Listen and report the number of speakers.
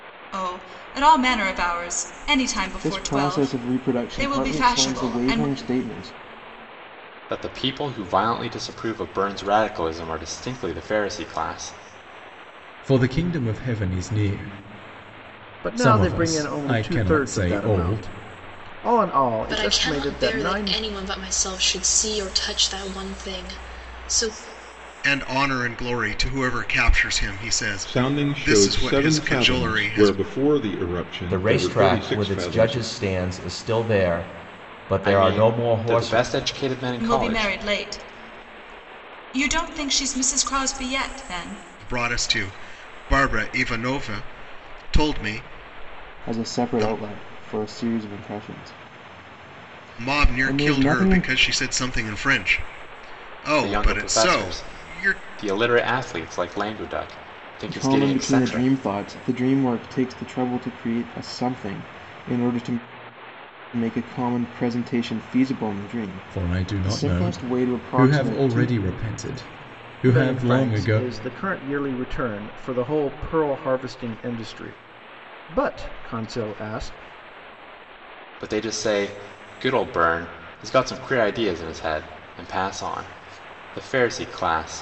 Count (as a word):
nine